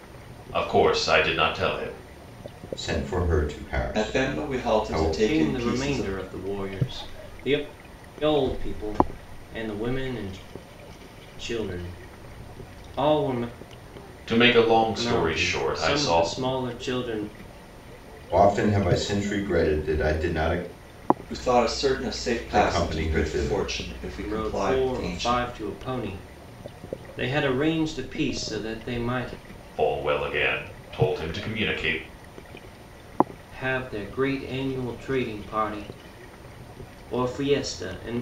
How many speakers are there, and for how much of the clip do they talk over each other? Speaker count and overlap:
four, about 15%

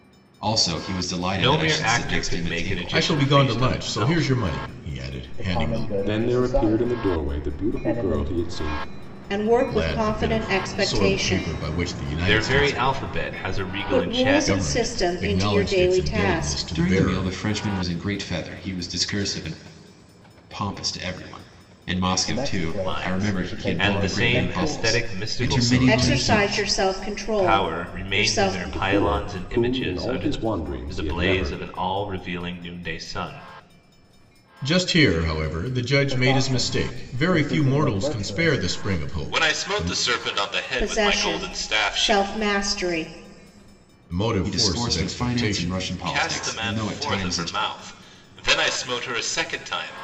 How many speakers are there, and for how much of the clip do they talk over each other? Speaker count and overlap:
six, about 55%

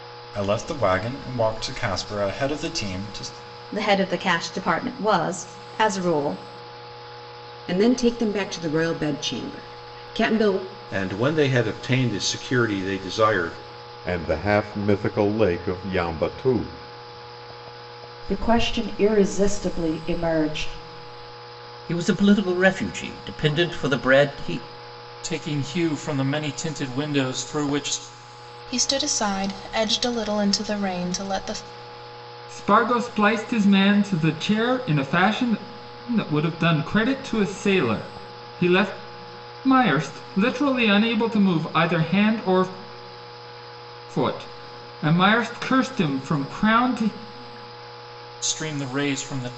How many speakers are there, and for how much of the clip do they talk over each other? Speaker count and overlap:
ten, no overlap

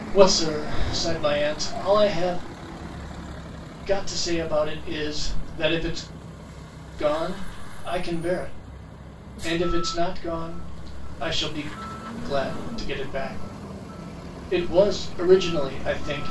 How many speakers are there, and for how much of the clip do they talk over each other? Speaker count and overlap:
one, no overlap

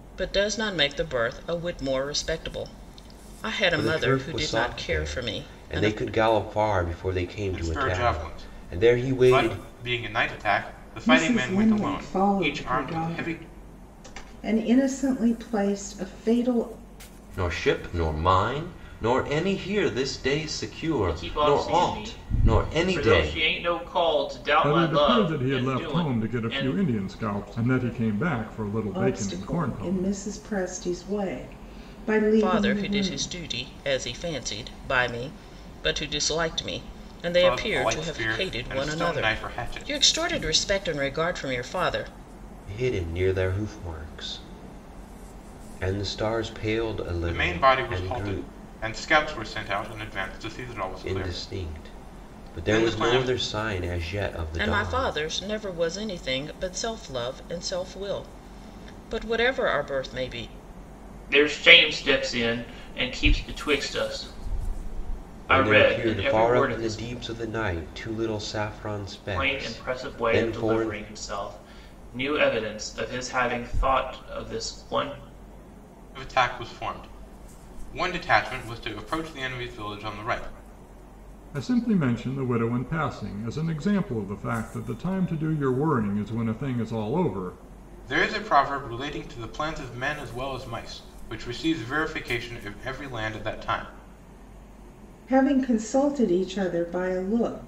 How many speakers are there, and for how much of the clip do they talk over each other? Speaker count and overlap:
seven, about 25%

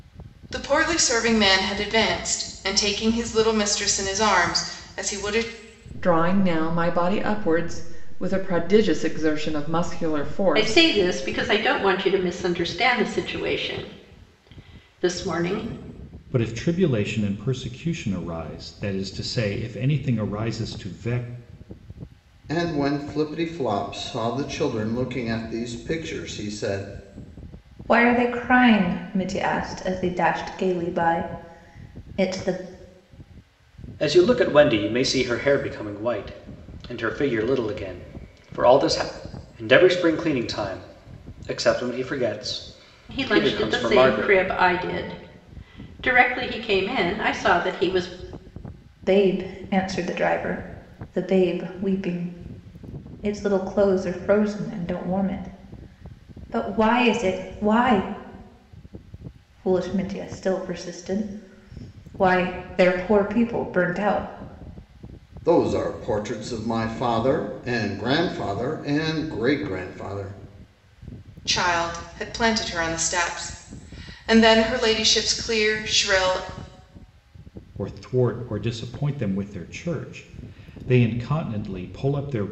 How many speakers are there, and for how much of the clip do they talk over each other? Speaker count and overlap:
seven, about 2%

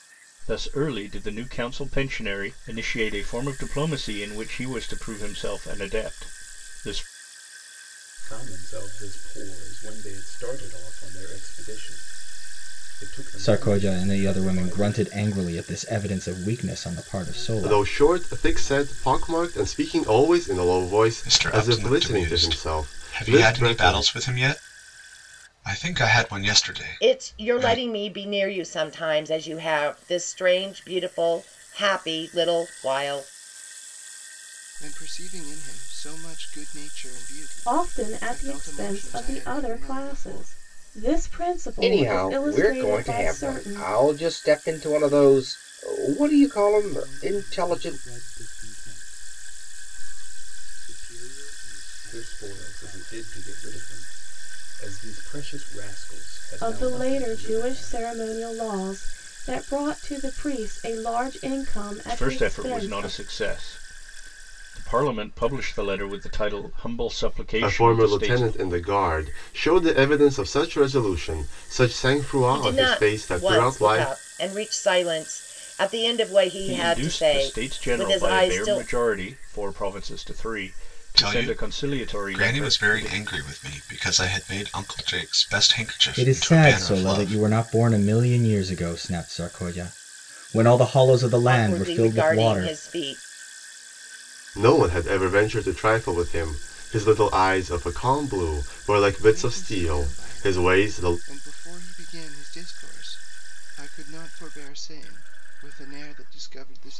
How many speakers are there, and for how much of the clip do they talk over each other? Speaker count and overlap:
ten, about 27%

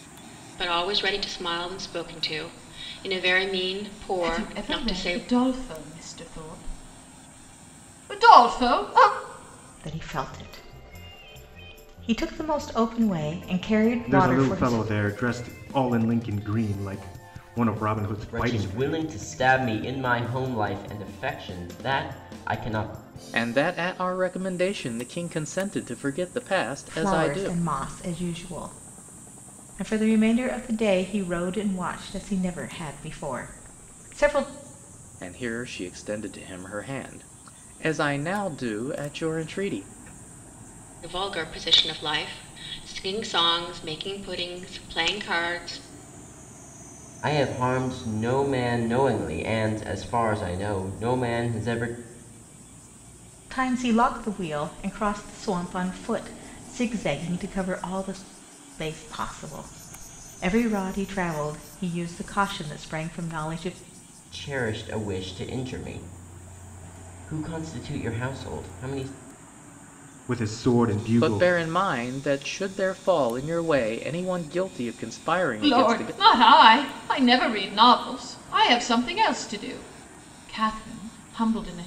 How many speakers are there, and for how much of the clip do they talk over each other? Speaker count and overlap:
six, about 5%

